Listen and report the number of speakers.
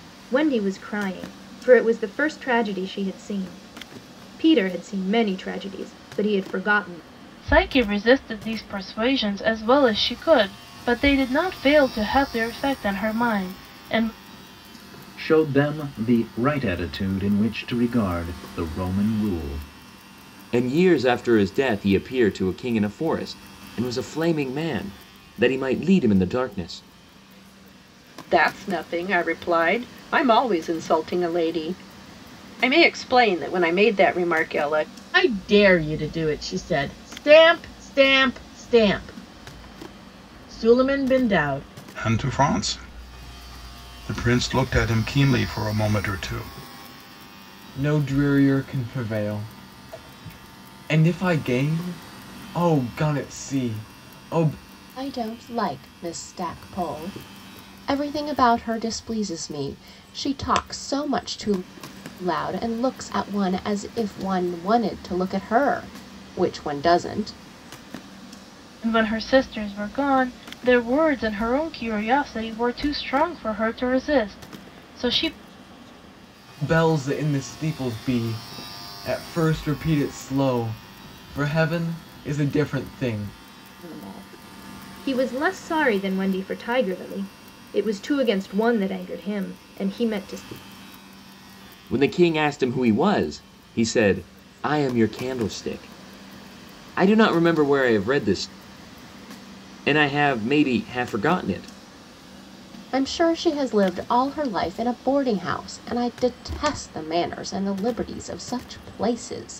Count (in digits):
9